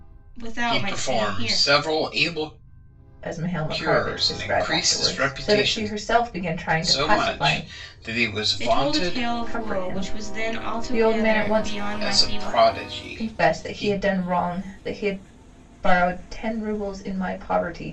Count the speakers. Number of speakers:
three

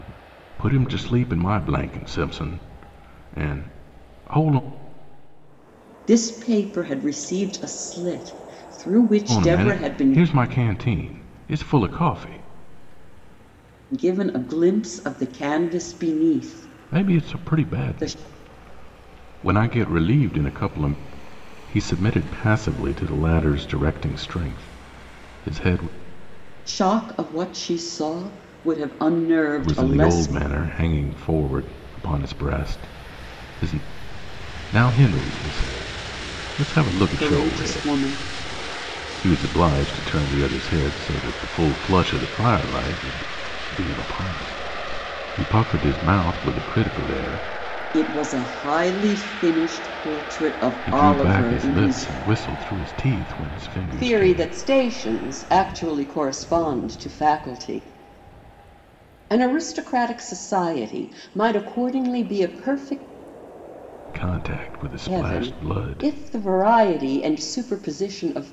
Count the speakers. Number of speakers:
two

